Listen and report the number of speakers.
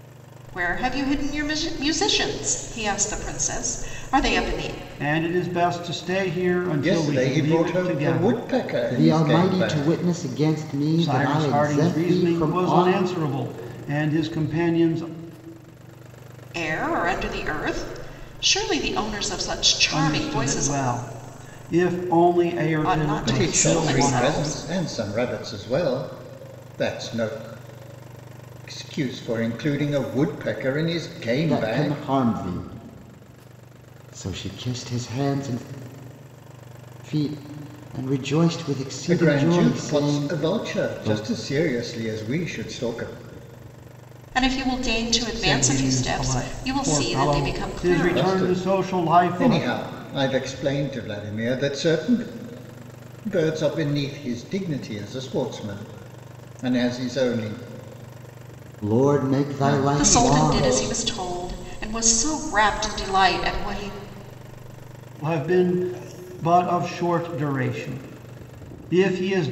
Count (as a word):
four